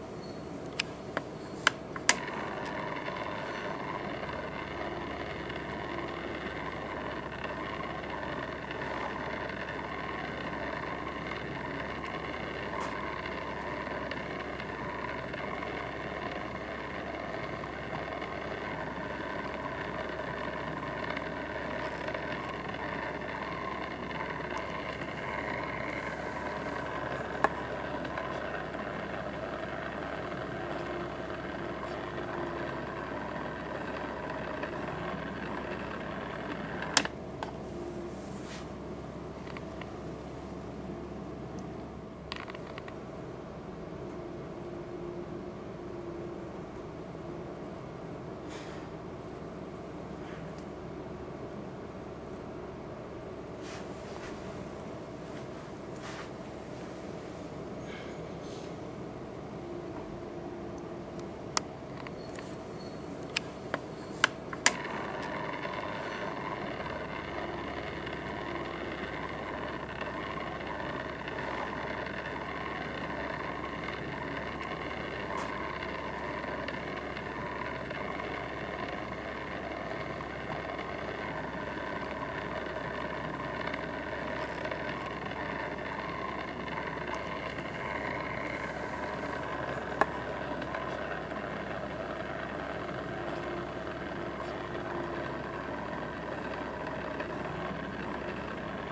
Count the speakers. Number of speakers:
zero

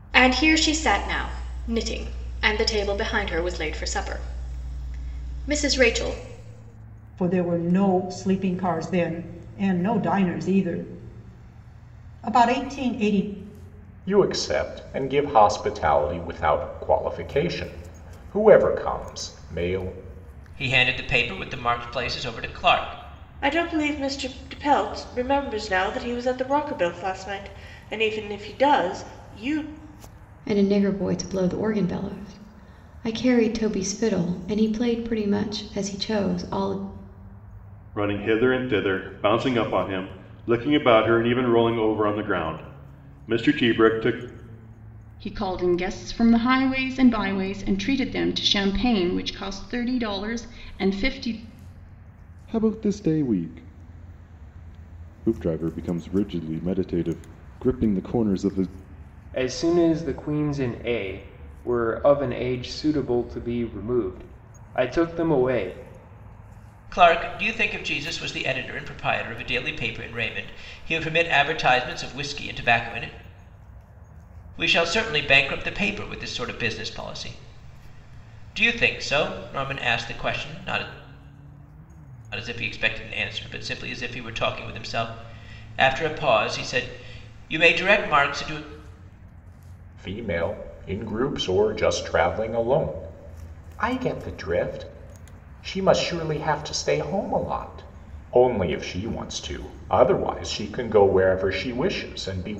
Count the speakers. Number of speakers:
ten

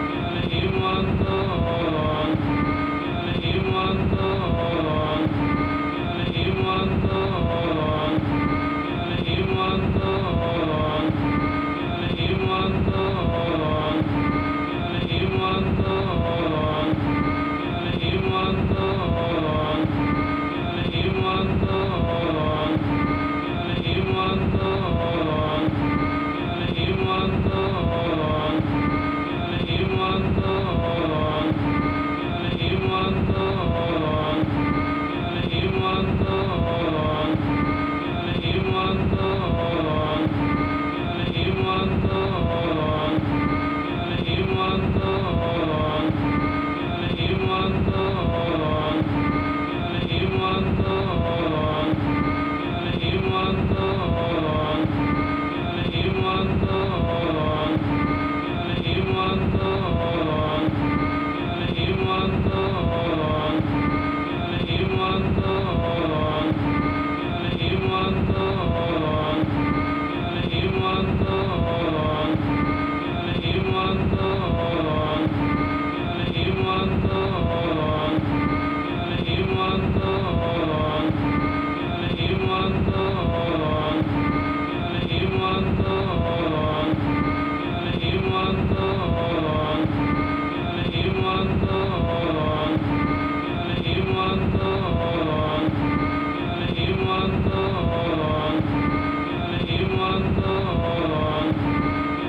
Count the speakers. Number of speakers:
zero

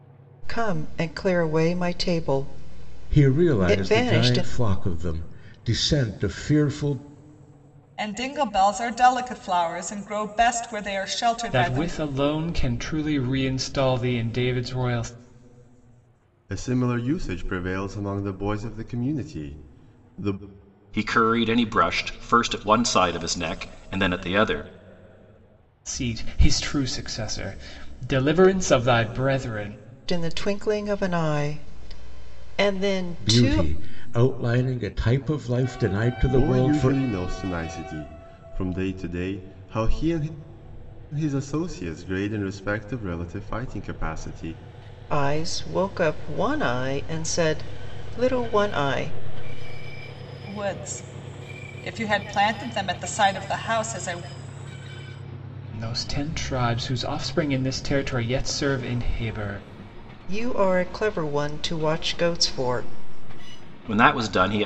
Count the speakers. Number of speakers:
six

